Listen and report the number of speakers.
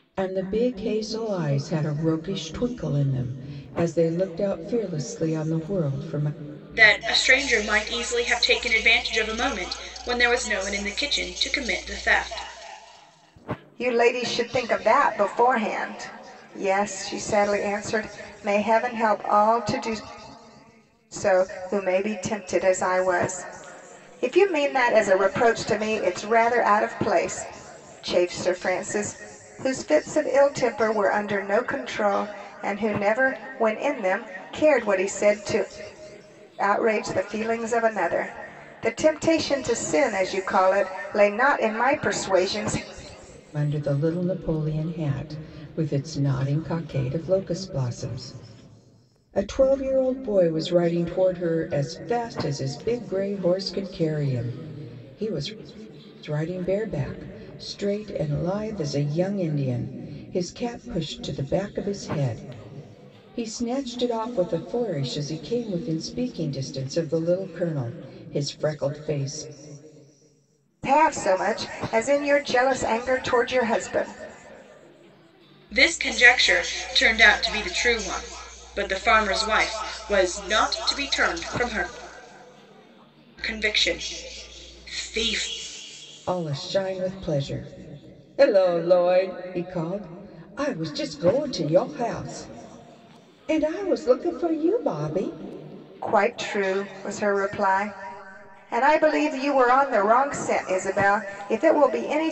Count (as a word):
three